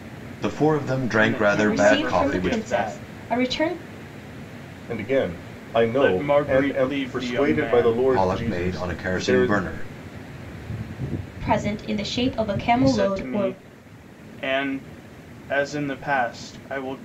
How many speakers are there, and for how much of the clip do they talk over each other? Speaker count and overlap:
4, about 36%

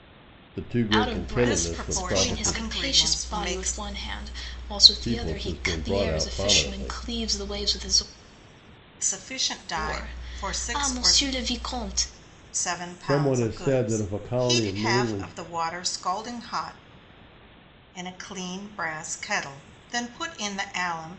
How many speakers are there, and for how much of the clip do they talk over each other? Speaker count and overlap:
3, about 41%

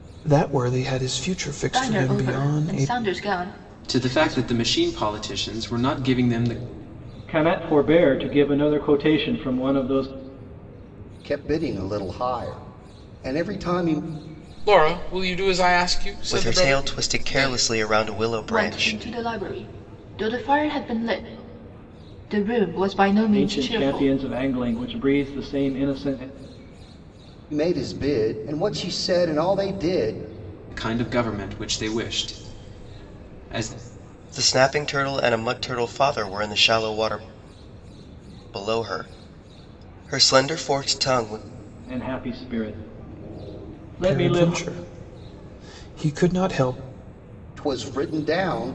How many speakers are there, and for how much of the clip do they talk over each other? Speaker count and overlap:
7, about 11%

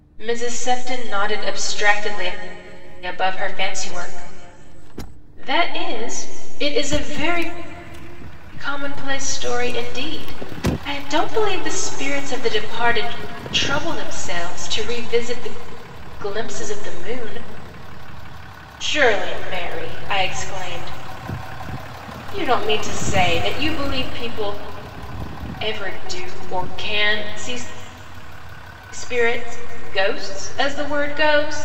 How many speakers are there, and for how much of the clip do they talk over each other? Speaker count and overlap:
1, no overlap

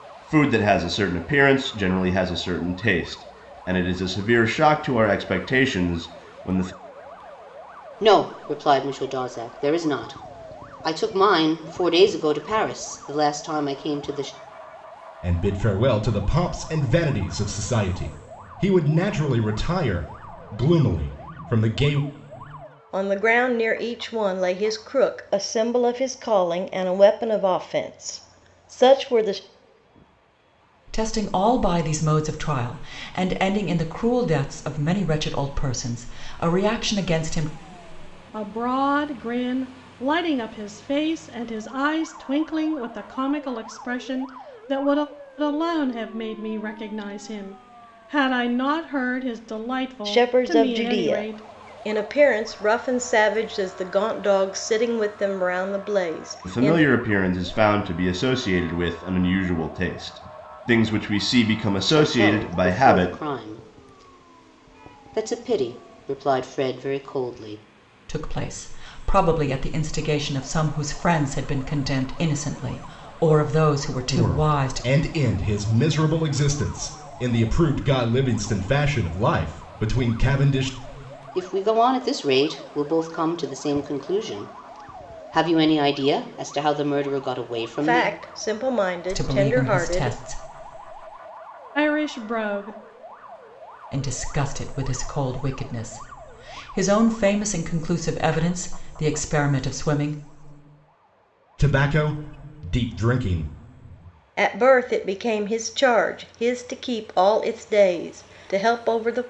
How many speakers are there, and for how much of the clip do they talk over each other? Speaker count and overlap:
6, about 5%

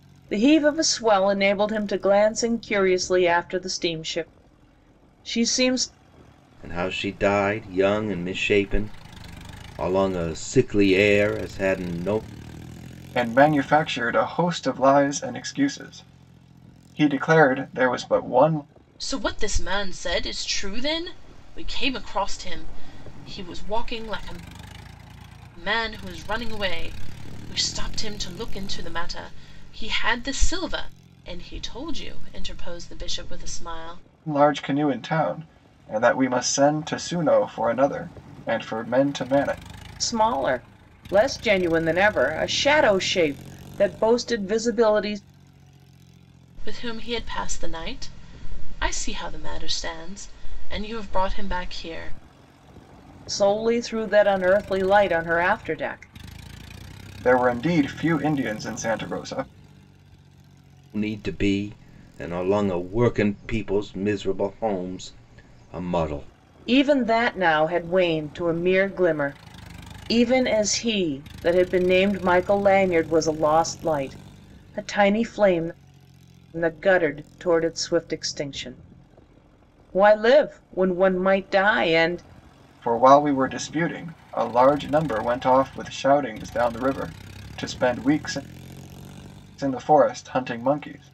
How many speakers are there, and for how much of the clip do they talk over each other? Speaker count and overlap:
4, no overlap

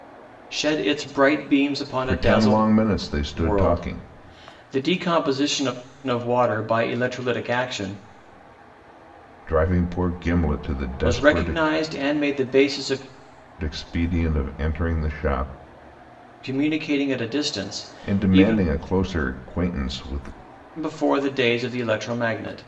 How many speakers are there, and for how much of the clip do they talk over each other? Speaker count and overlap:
2, about 12%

